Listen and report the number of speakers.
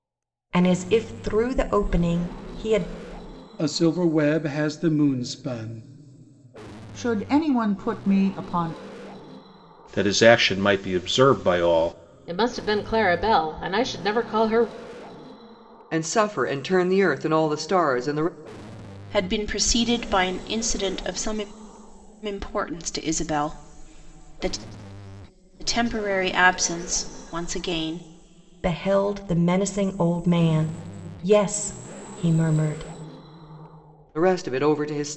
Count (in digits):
7